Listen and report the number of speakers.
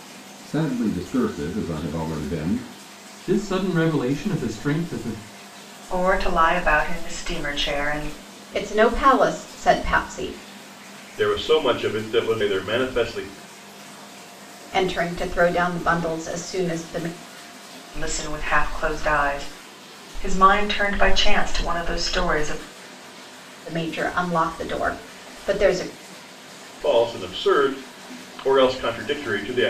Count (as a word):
five